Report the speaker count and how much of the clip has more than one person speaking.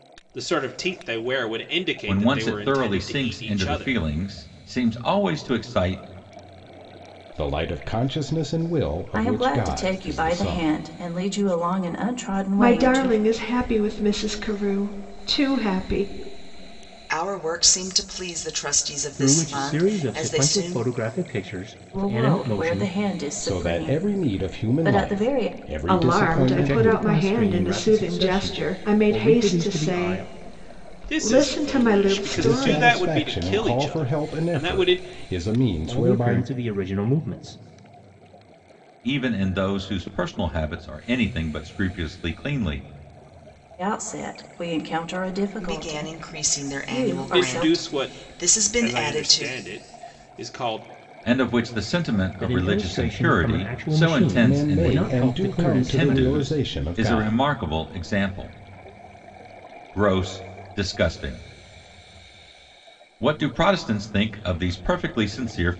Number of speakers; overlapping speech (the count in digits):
7, about 41%